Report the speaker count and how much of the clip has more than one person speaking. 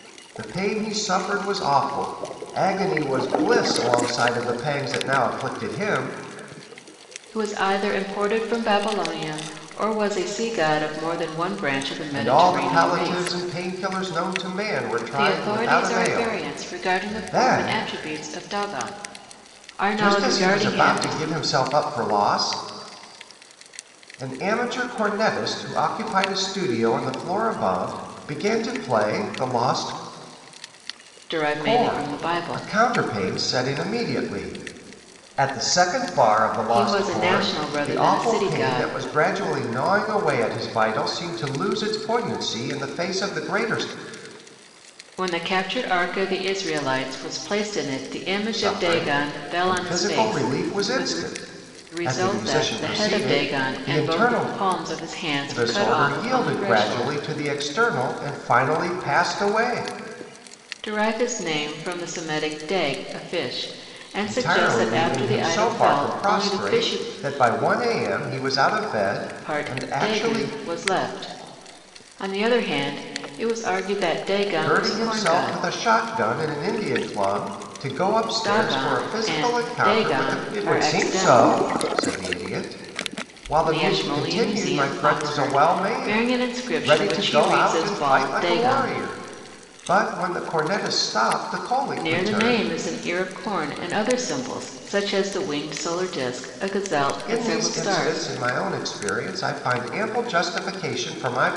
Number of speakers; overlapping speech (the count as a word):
two, about 30%